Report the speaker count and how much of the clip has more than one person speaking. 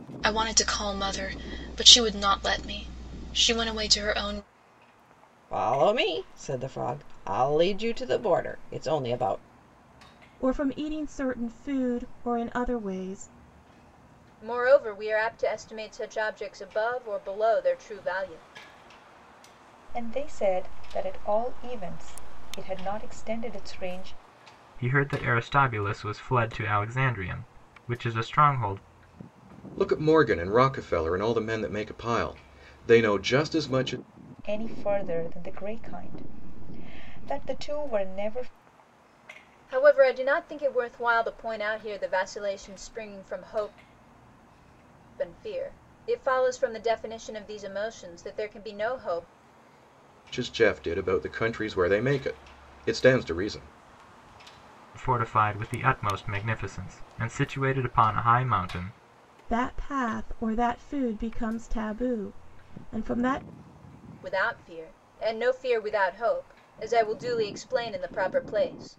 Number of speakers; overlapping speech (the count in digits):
7, no overlap